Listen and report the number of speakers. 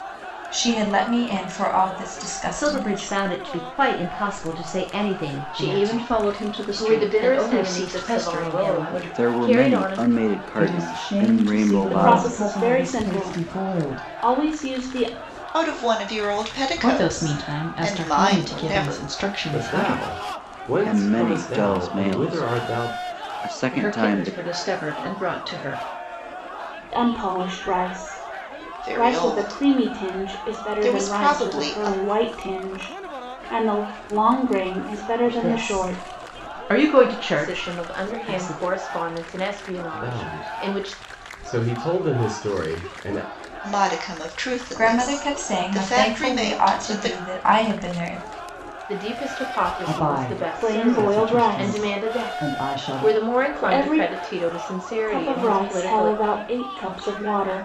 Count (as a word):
ten